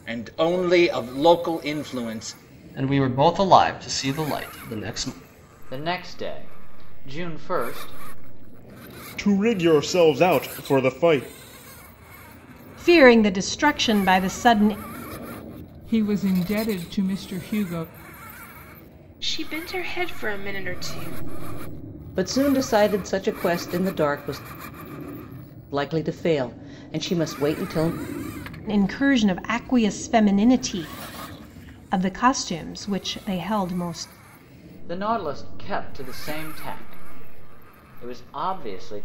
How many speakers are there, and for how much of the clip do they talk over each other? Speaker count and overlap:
8, no overlap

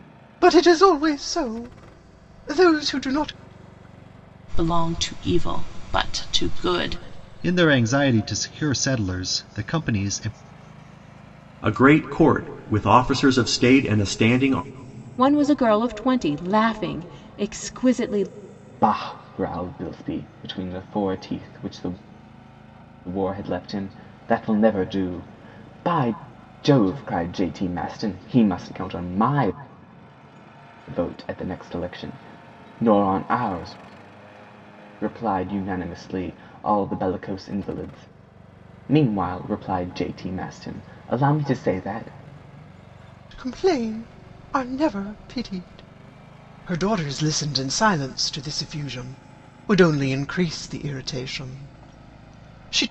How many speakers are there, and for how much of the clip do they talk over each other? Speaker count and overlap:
6, no overlap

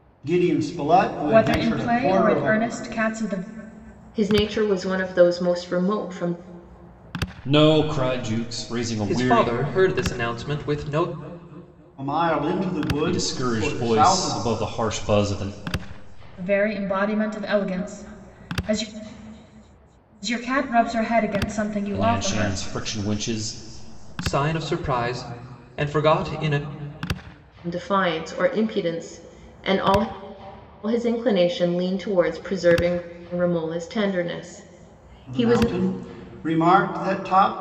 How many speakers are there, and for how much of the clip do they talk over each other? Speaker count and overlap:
5, about 11%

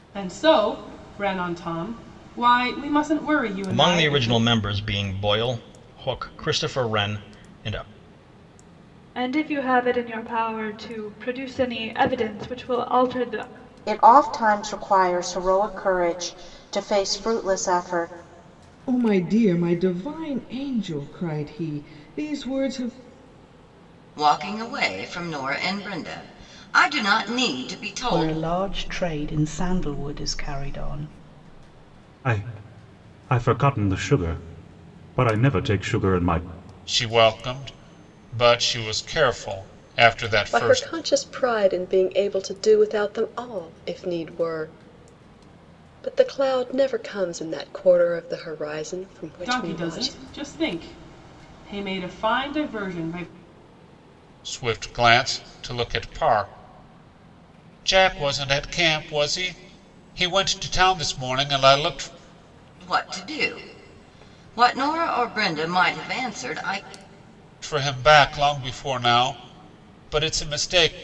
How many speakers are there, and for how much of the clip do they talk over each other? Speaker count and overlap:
10, about 3%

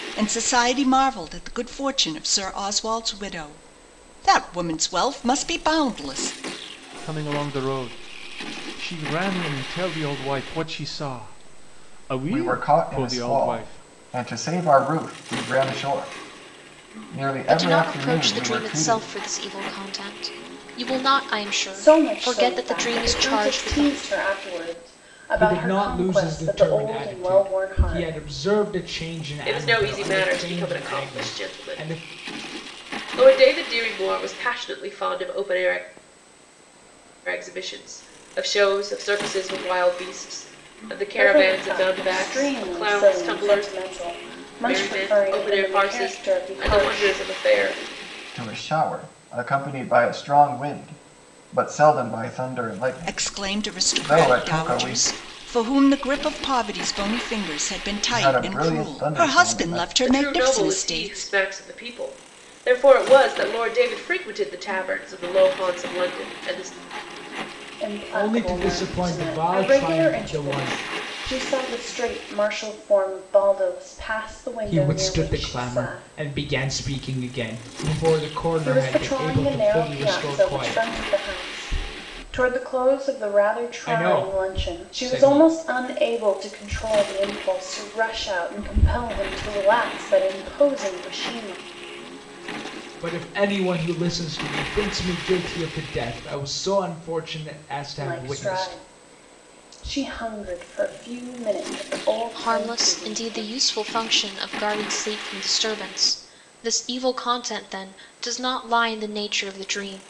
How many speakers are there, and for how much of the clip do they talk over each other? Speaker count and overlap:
7, about 29%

